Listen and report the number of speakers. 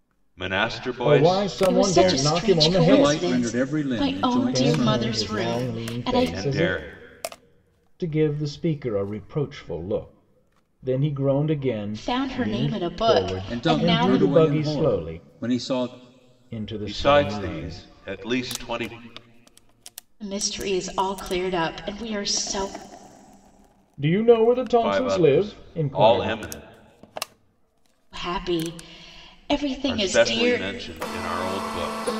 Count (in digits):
4